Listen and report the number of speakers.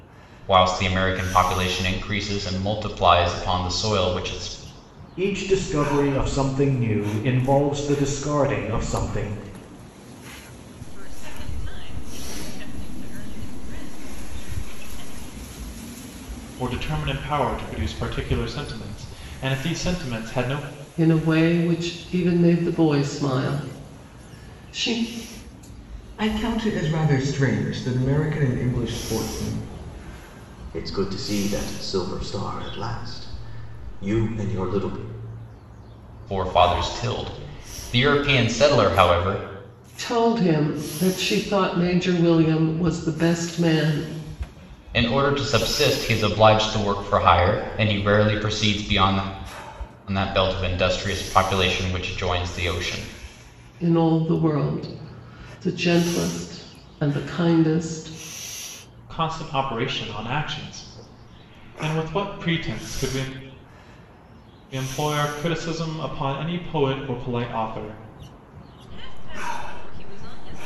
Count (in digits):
7